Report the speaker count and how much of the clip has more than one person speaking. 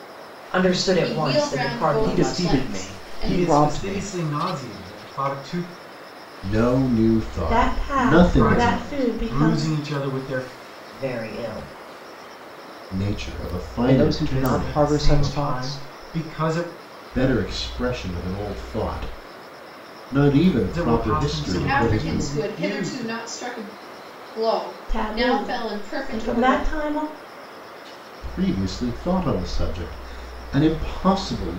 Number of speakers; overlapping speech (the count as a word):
six, about 37%